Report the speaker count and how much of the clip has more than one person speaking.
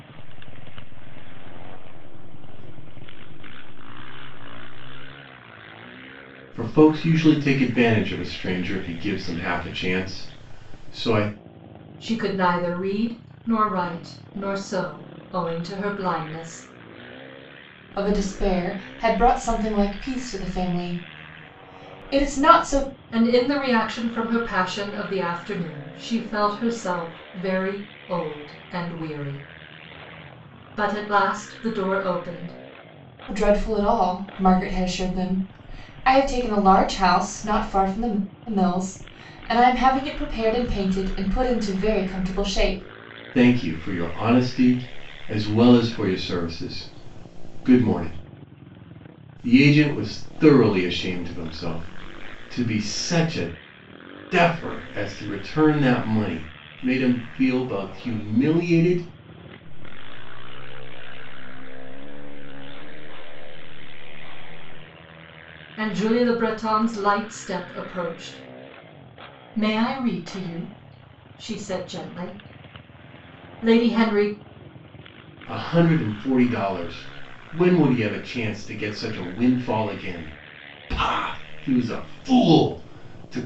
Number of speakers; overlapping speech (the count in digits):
4, no overlap